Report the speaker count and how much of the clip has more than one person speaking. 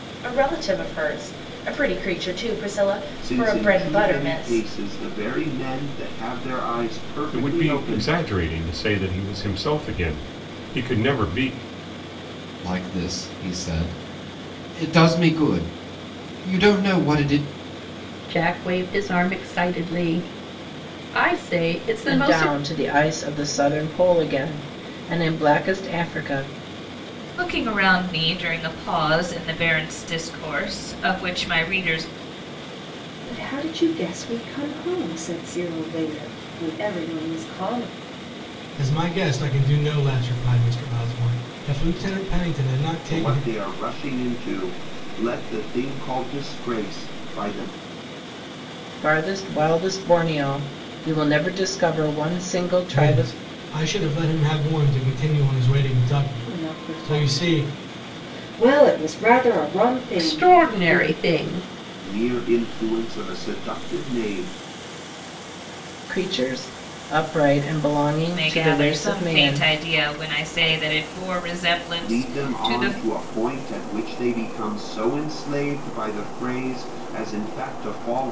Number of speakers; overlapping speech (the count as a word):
nine, about 10%